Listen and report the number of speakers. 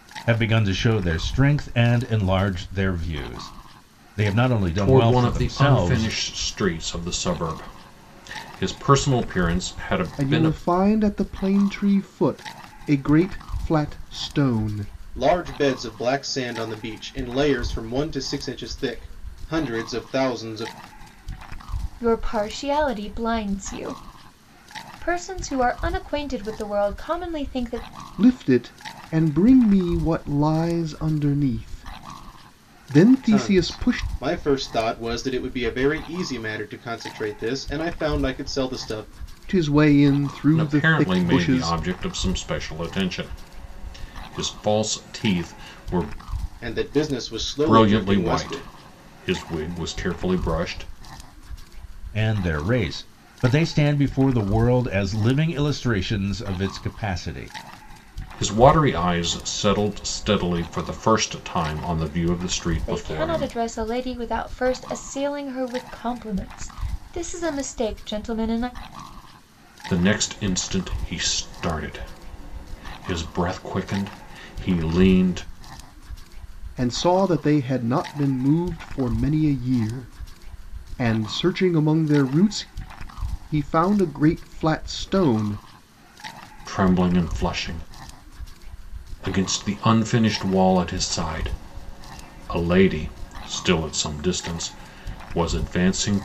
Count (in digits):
5